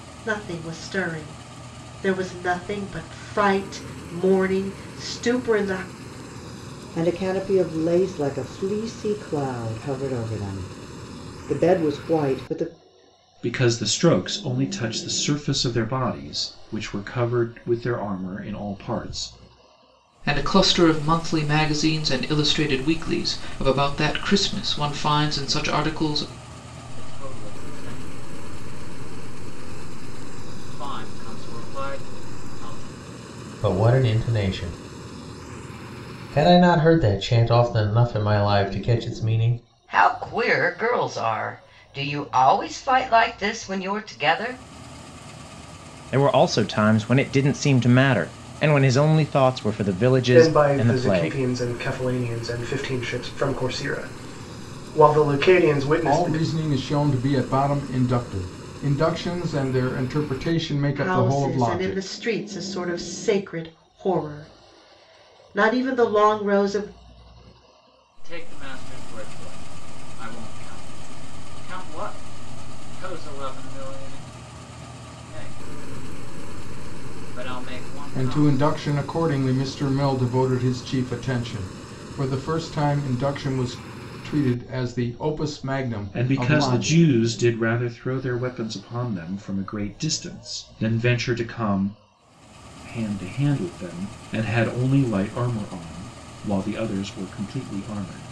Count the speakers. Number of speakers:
10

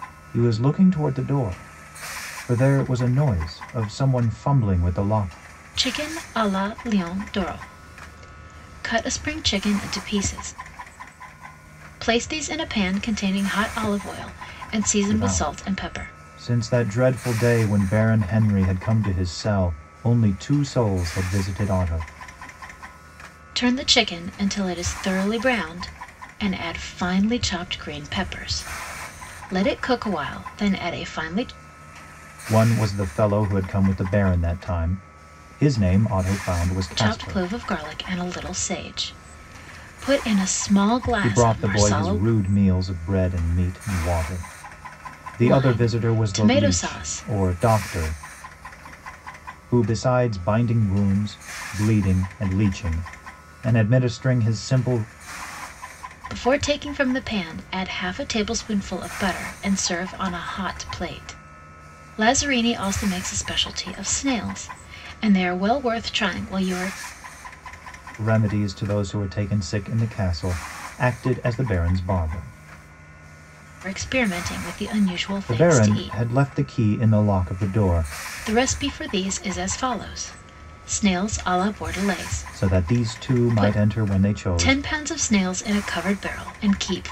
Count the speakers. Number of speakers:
2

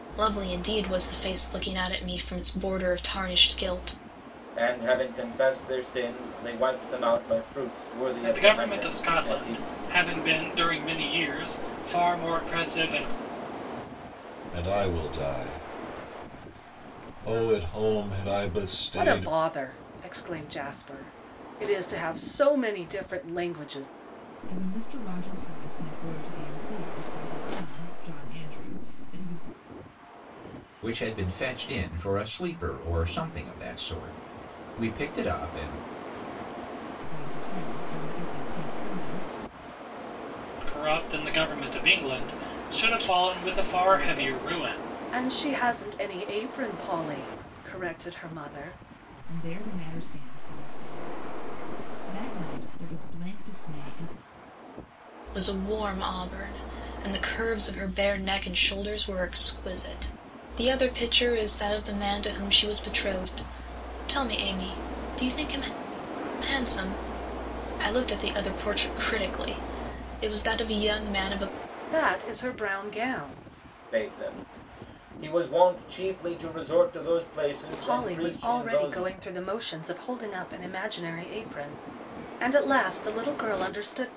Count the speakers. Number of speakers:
7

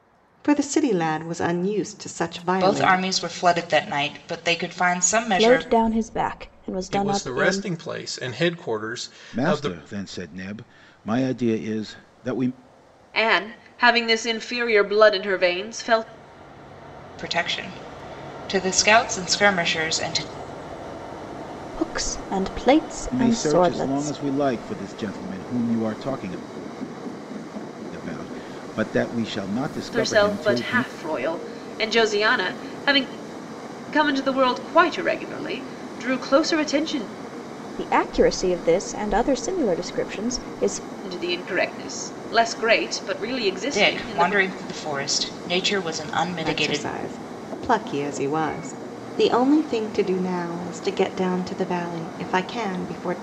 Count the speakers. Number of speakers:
6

